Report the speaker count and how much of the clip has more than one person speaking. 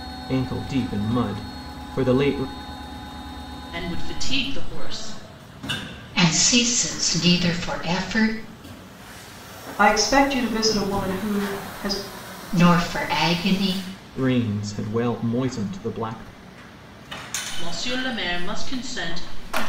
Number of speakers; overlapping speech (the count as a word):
four, no overlap